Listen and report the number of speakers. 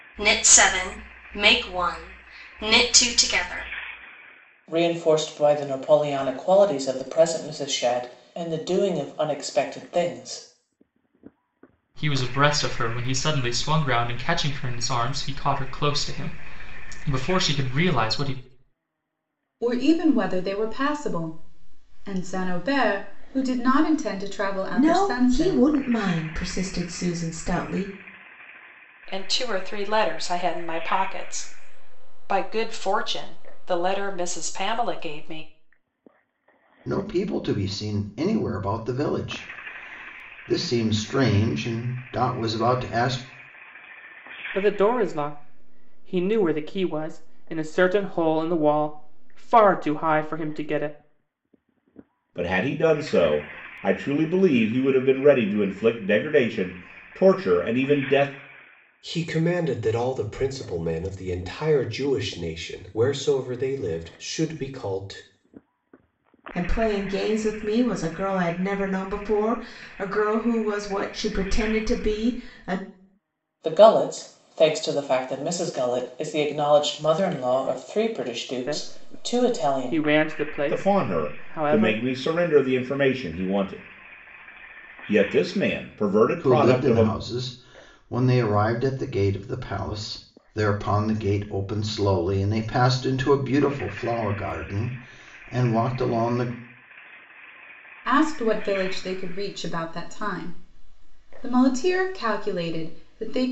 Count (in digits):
10